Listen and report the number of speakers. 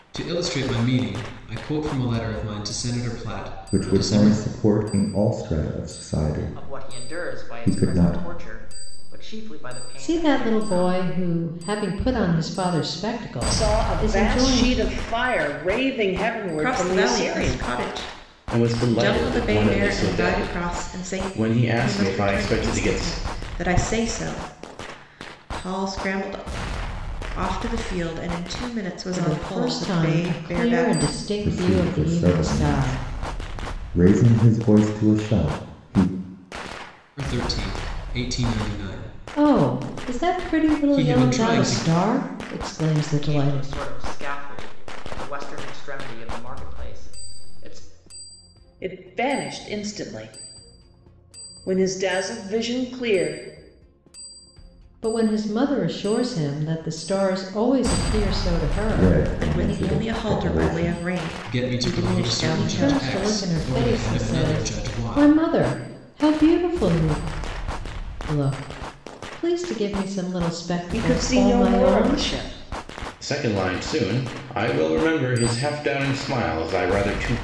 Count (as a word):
seven